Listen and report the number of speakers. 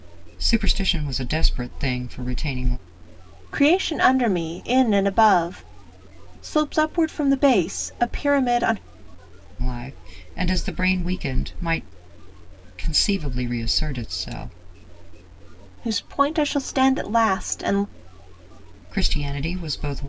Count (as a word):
two